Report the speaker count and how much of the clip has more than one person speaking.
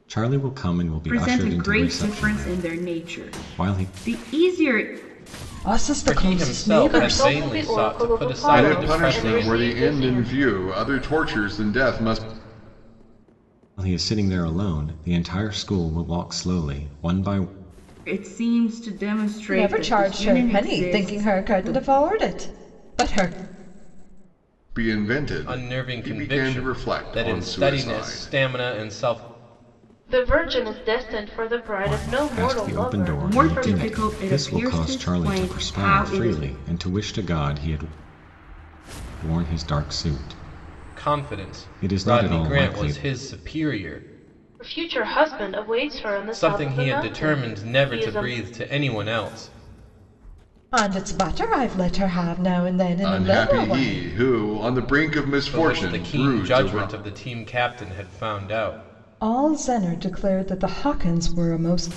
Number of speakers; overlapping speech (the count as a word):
six, about 39%